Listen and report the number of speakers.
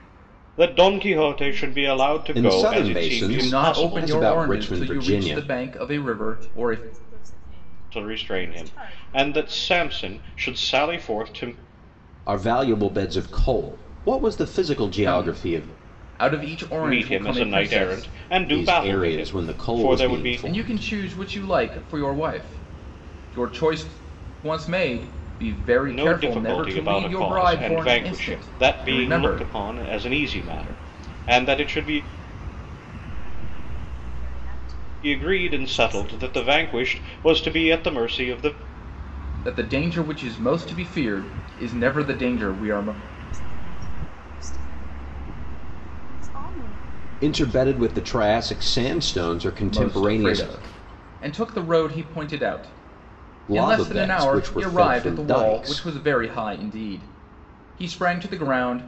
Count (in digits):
4